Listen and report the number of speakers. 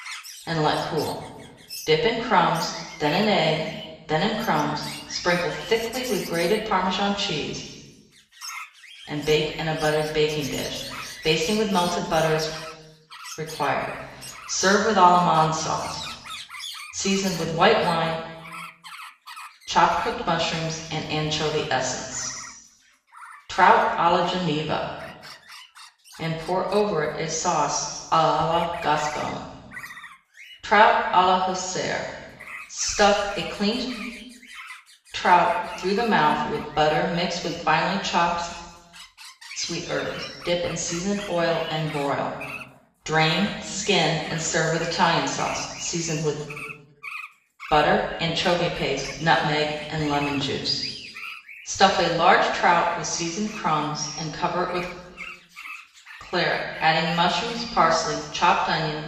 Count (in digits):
1